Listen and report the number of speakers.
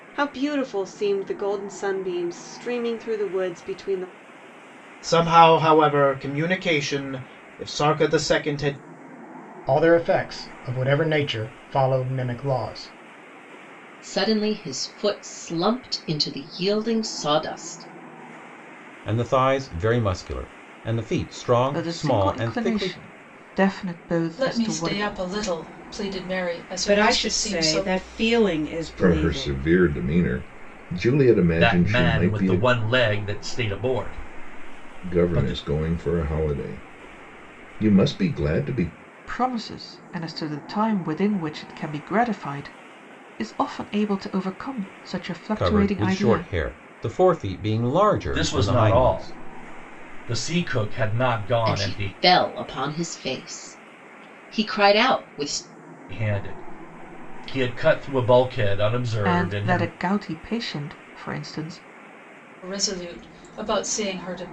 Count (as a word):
ten